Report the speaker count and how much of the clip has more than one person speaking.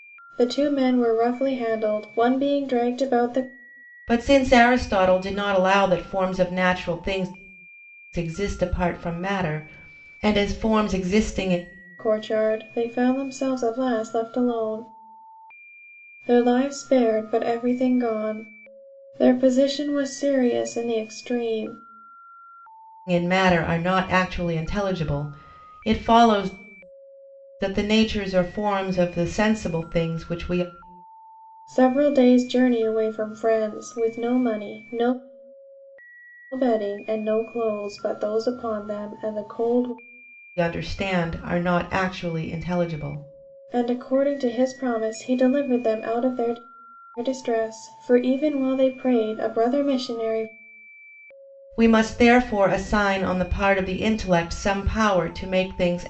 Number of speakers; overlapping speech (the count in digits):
2, no overlap